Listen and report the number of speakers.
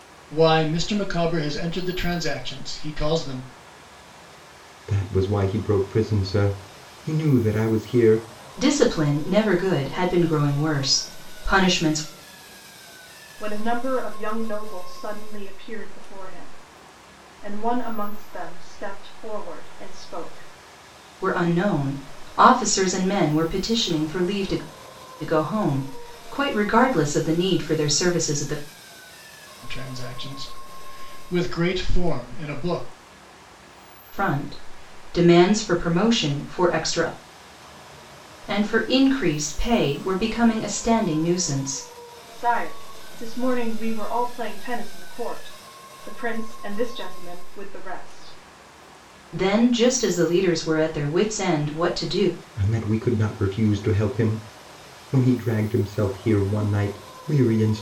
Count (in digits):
4